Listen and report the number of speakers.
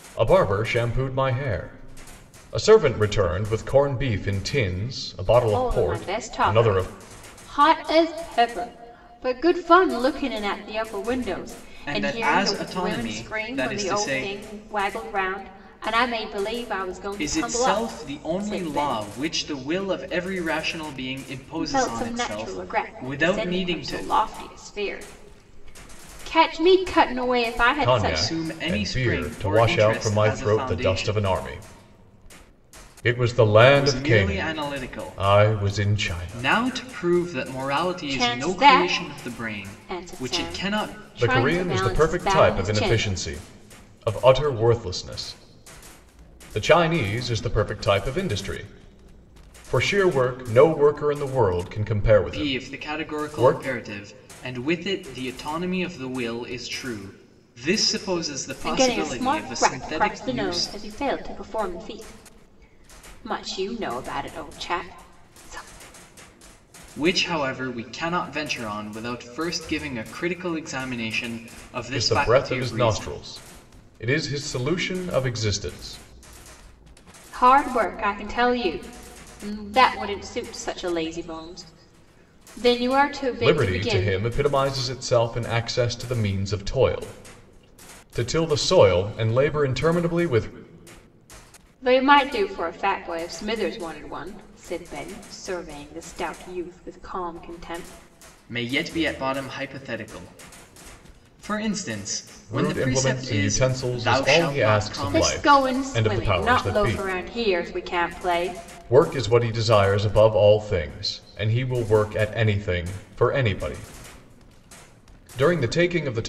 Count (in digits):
3